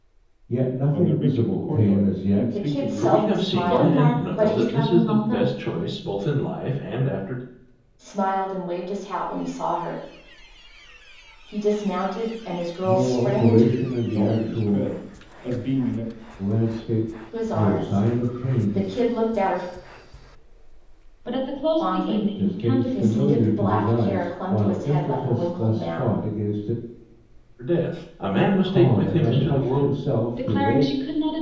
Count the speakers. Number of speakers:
5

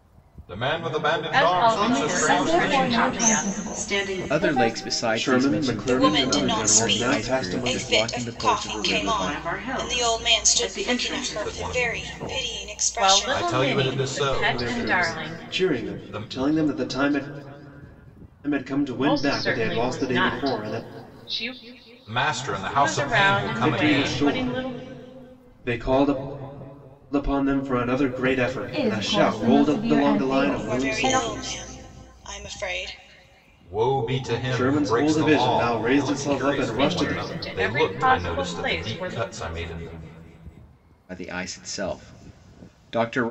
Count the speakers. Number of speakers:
7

